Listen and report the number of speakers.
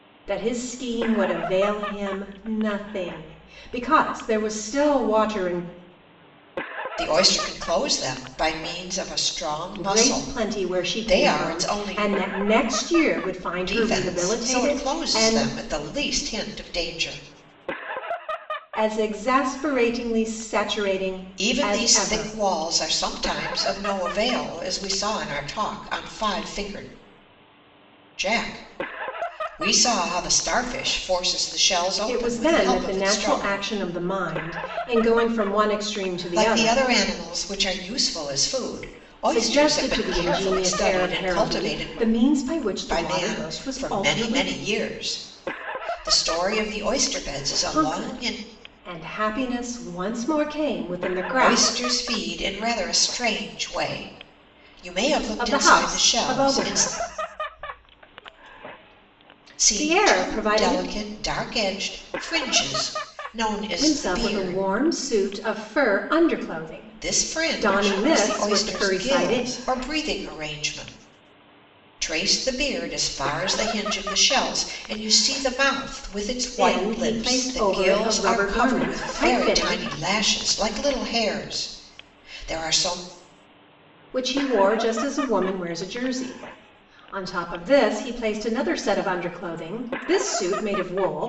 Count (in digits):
2